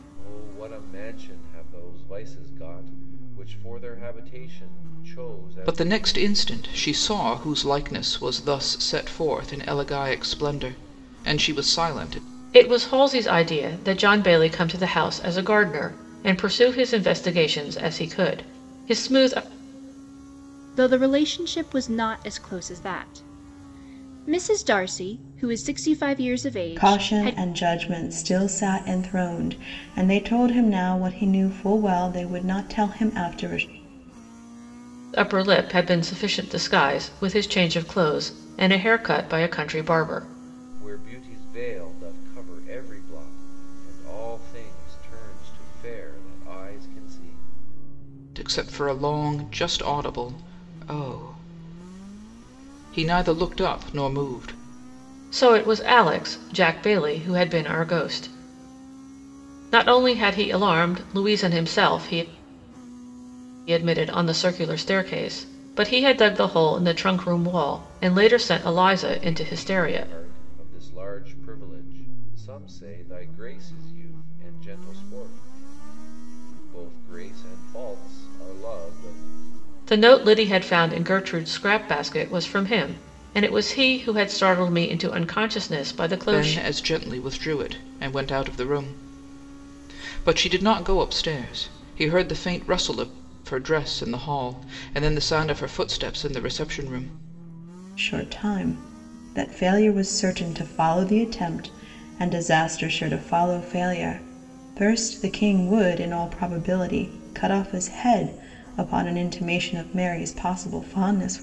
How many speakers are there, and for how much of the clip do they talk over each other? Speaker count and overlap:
5, about 2%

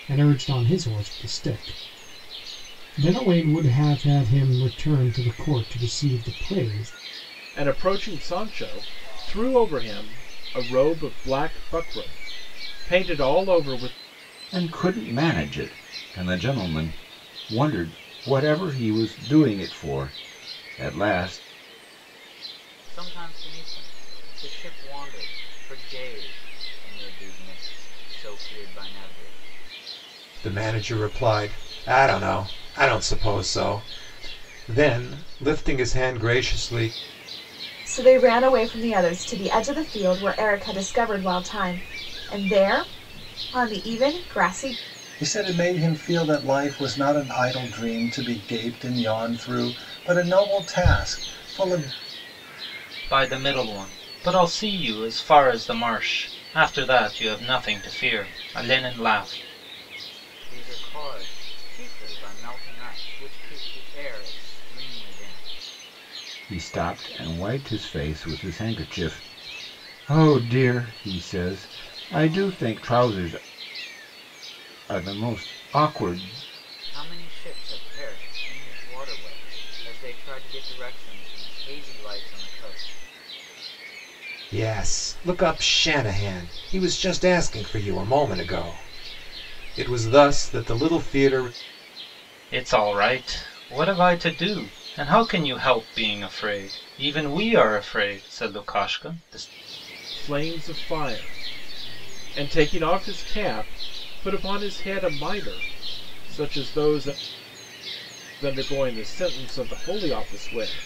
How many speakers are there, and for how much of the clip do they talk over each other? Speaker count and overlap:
8, no overlap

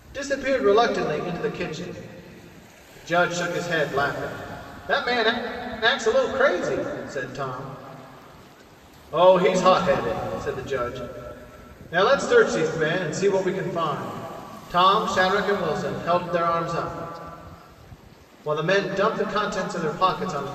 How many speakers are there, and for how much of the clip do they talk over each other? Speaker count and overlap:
1, no overlap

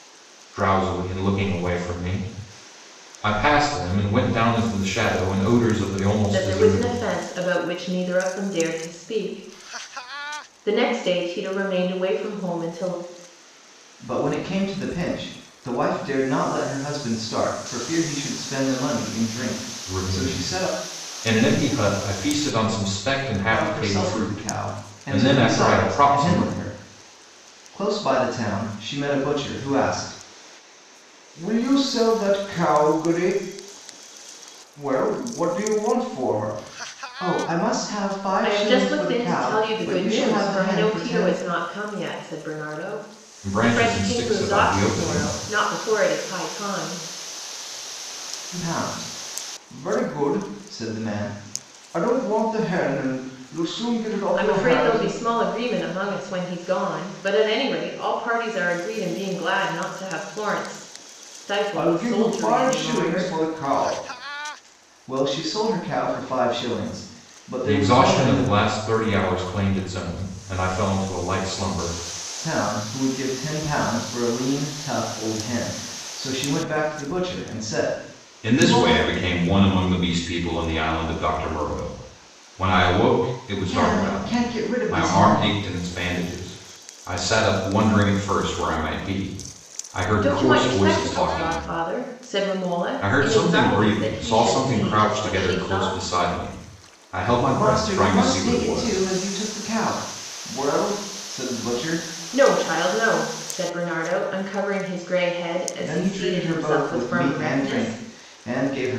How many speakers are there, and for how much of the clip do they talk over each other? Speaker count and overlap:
3, about 21%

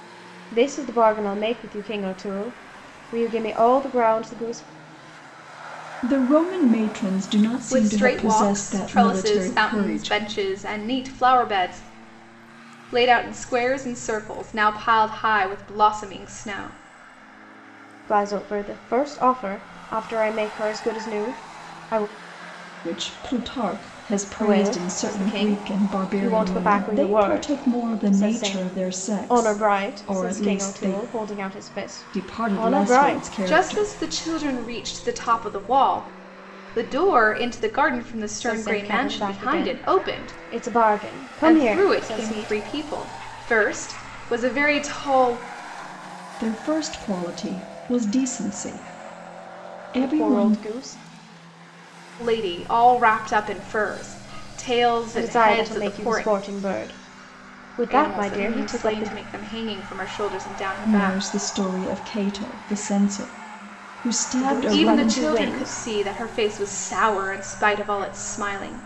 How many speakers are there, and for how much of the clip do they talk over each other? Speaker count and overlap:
3, about 27%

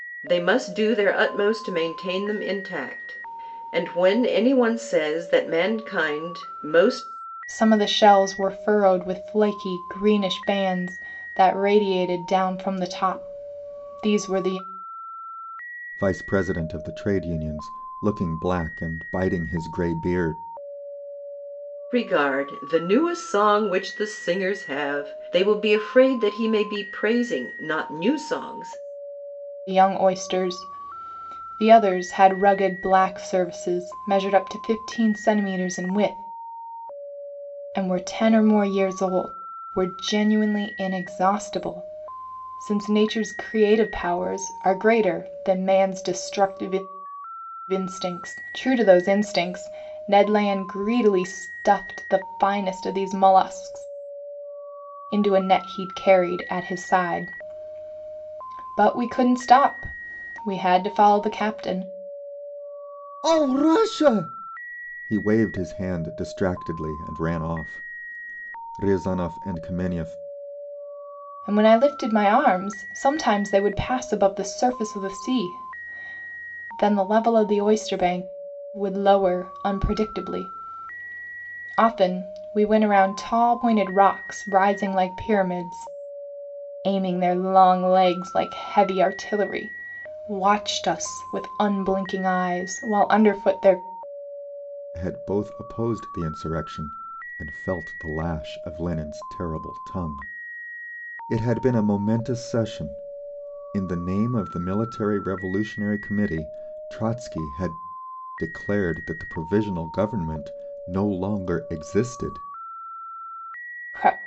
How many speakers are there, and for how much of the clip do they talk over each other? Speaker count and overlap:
3, no overlap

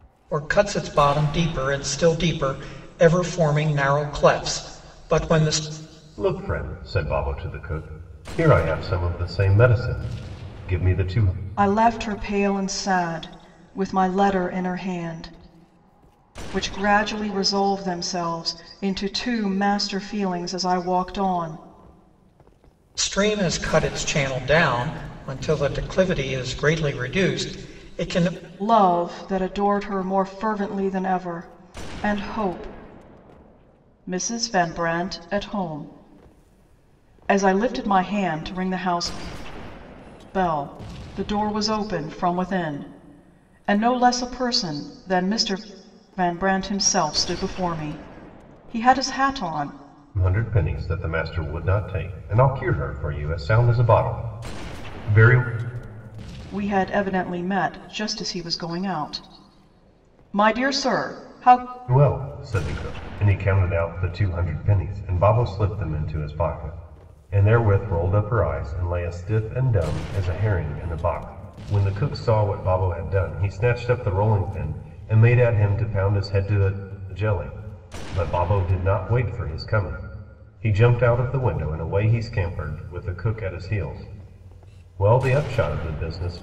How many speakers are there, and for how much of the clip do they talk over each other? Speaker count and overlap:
3, no overlap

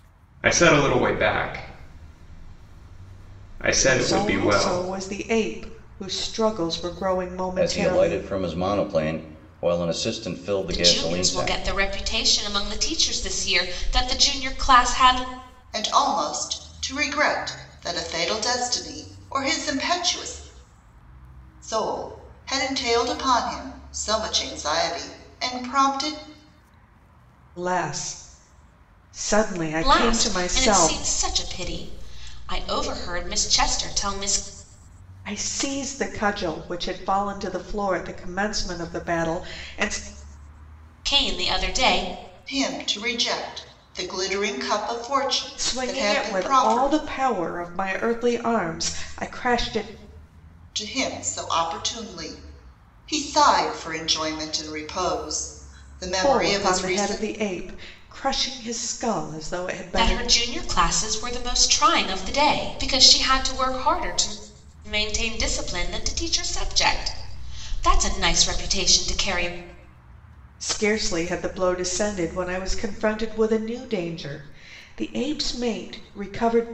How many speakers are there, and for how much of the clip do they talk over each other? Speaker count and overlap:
5, about 9%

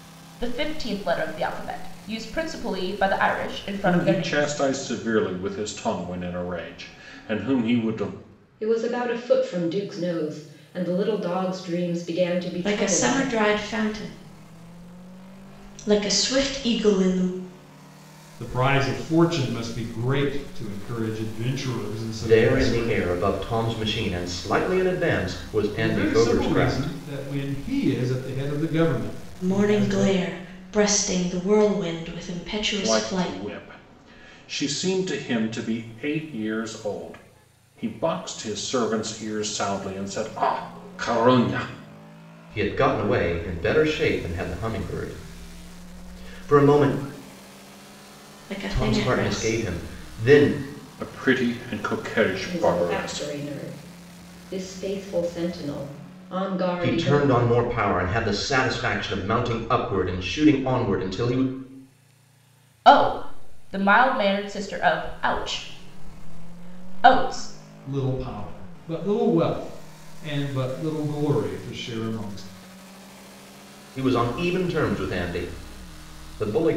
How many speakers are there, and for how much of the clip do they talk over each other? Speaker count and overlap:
6, about 10%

